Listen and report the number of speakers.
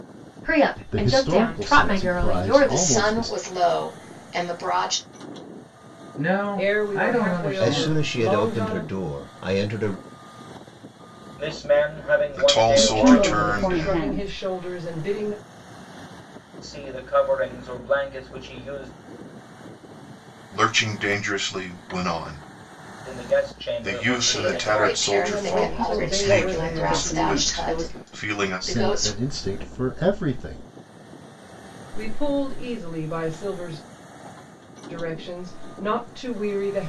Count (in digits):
9